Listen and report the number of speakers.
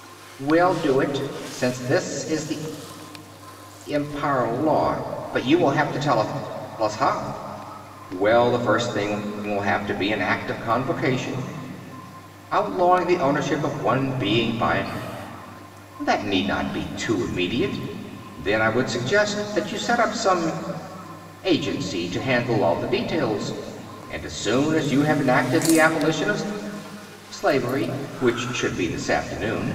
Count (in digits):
1